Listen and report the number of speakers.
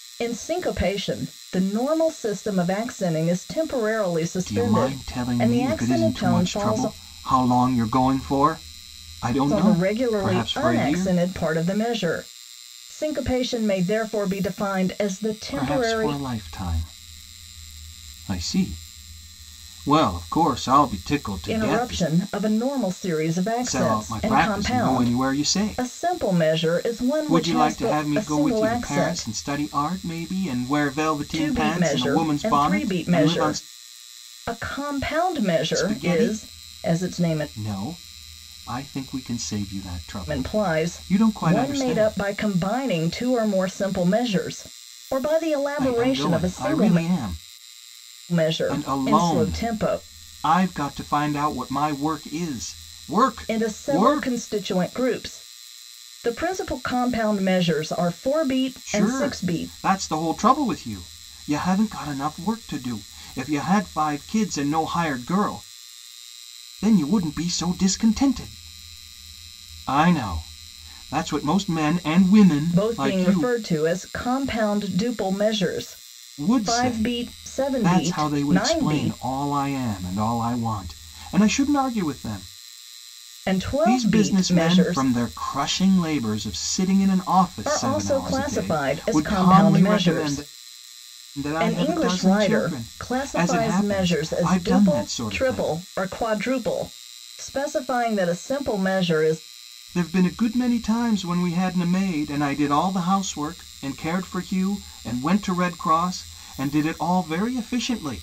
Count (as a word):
two